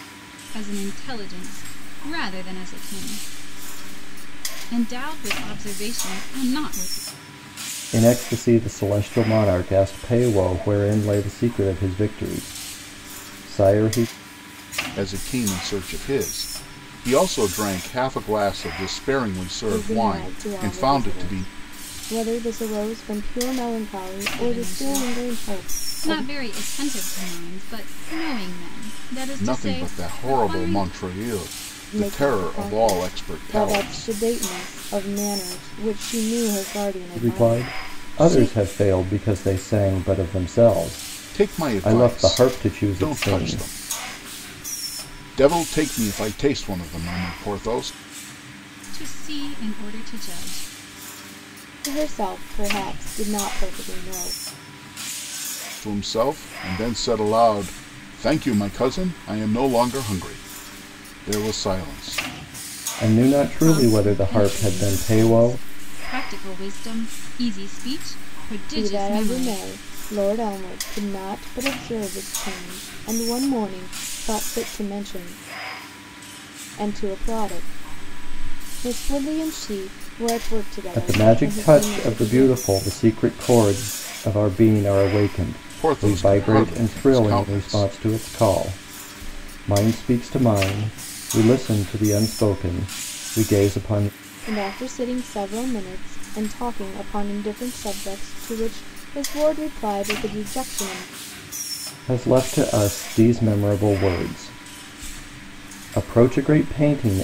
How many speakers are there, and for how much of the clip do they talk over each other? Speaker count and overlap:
4, about 17%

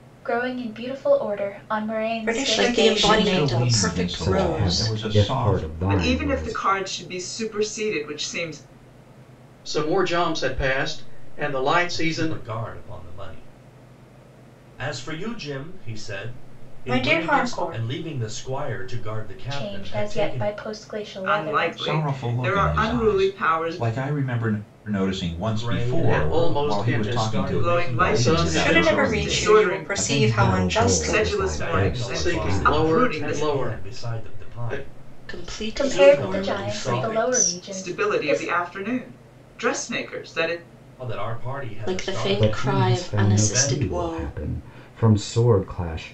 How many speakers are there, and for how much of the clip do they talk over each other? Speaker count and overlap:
8, about 54%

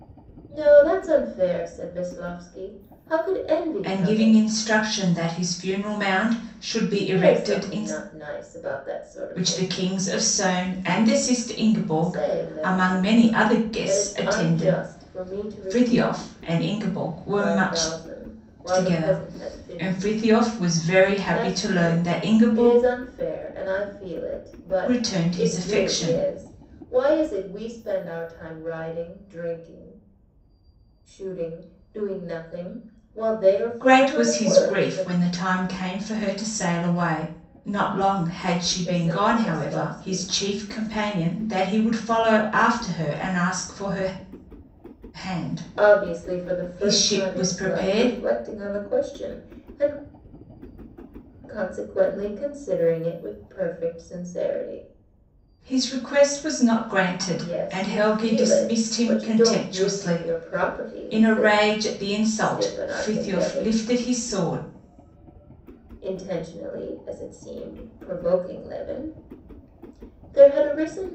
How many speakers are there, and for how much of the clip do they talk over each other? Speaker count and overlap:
2, about 33%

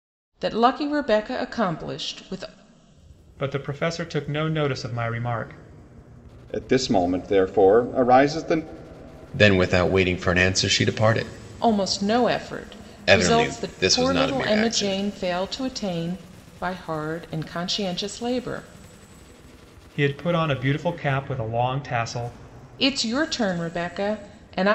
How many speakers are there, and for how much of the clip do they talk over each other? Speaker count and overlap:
4, about 8%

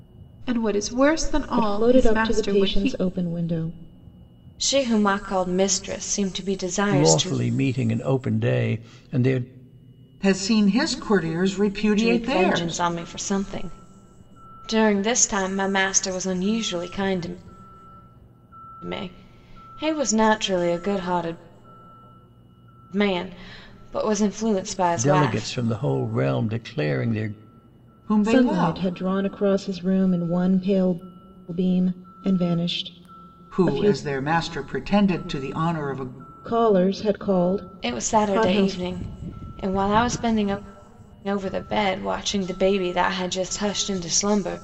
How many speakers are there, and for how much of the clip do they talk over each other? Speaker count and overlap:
5, about 13%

